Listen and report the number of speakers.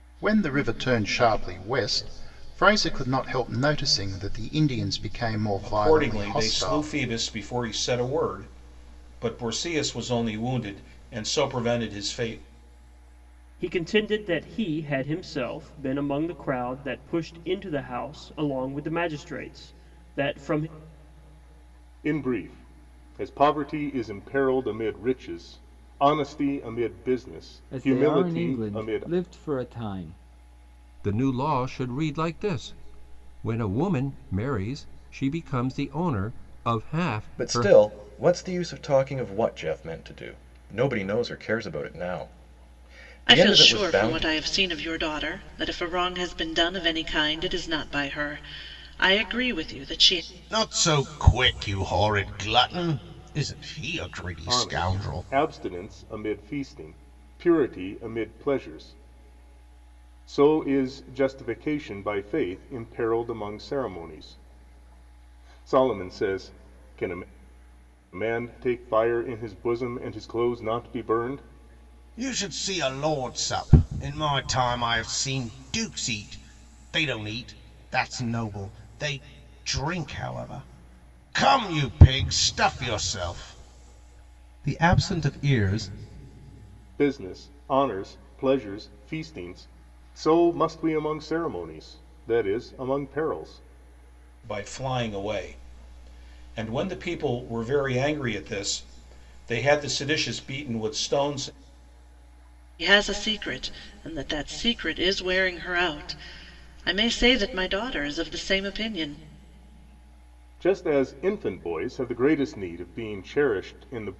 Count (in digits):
9